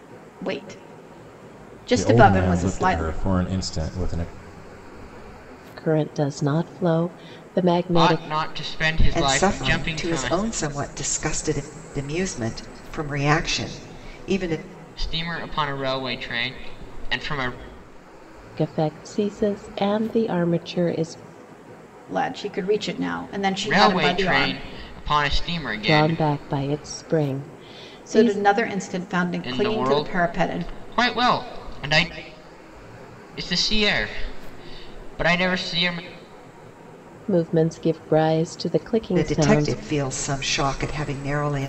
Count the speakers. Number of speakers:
five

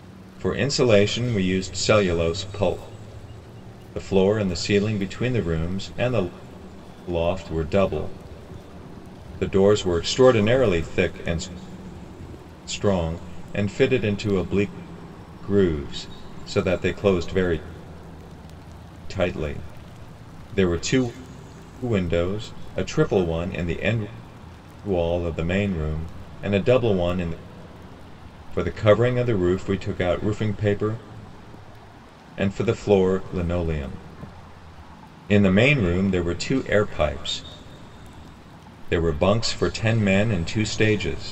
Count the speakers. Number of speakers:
one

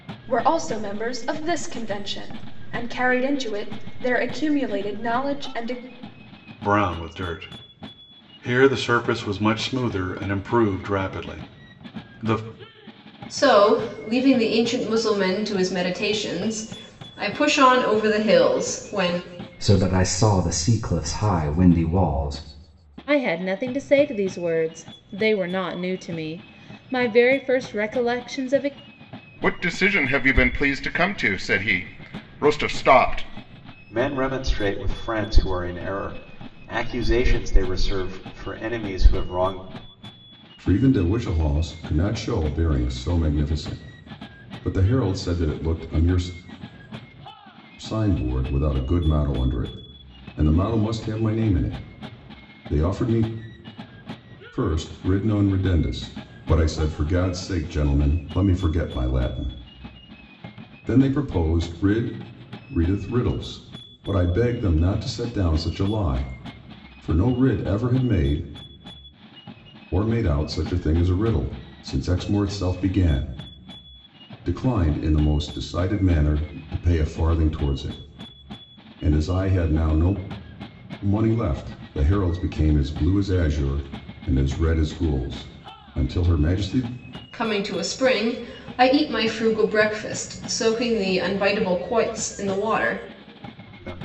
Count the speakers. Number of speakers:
eight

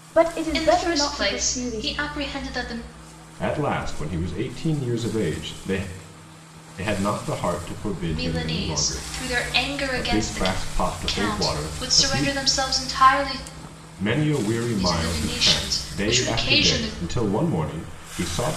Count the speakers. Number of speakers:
three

